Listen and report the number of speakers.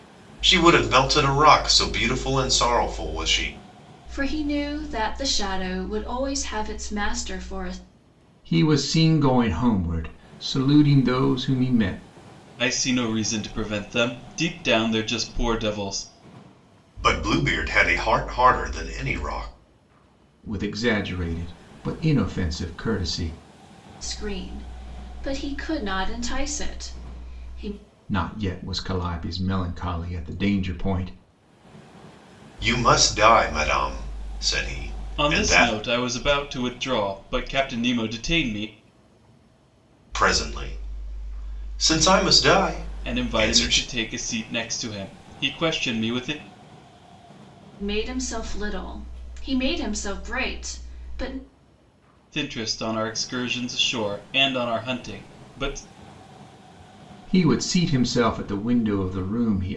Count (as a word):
four